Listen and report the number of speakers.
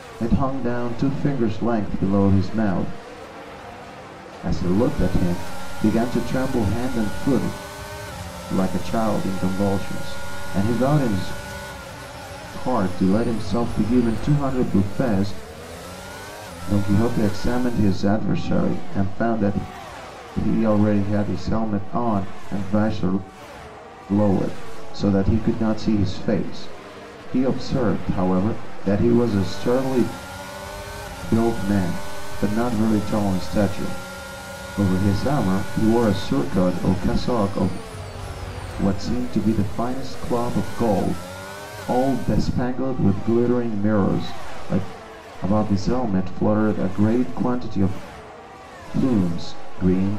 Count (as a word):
one